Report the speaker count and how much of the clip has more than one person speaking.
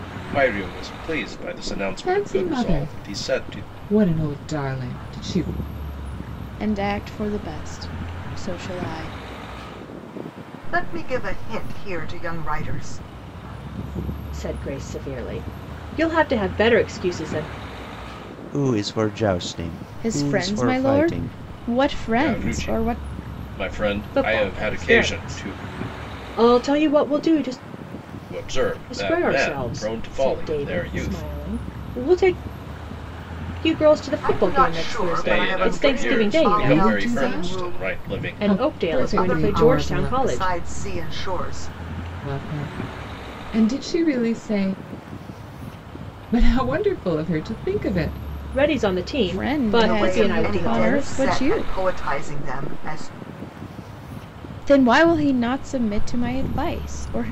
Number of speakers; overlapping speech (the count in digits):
6, about 29%